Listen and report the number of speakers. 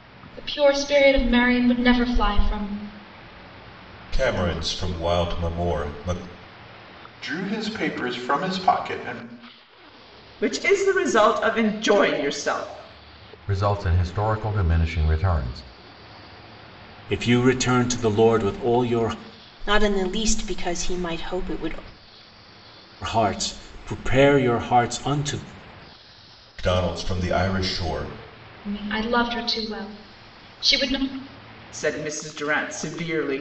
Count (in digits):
7